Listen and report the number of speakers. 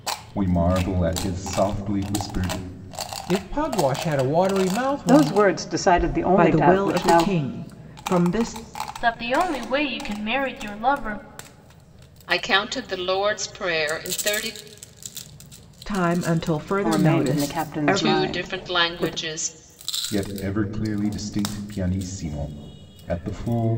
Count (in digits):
6